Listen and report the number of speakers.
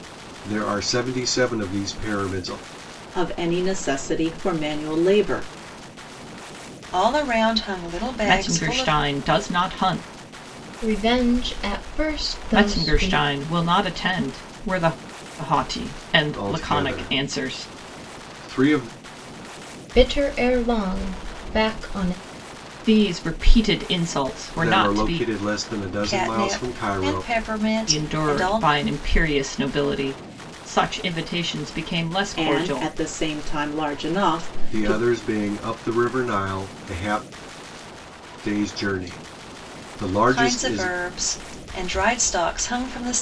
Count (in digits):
5